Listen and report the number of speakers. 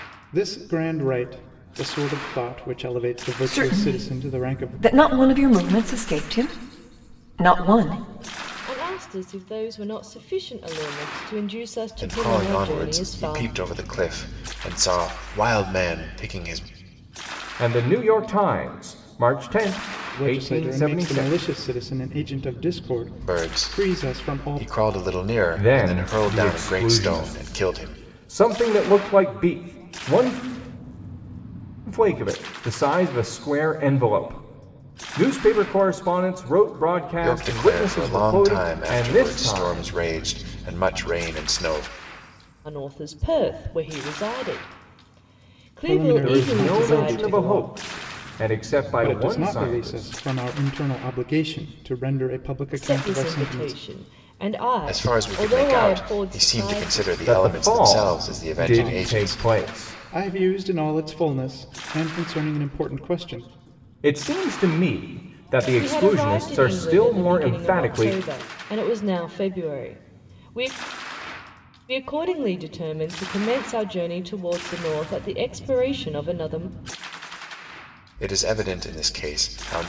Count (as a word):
five